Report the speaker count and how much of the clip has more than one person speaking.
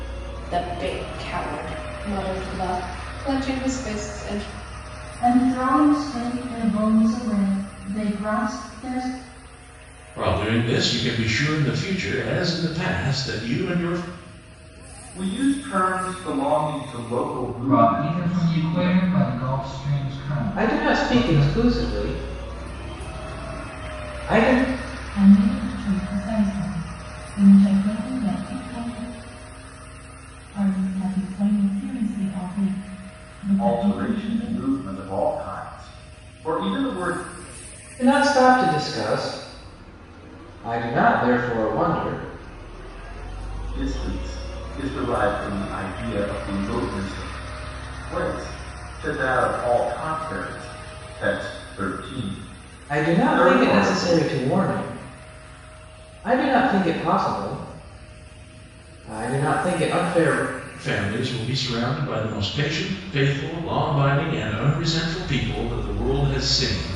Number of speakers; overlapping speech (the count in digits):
7, about 7%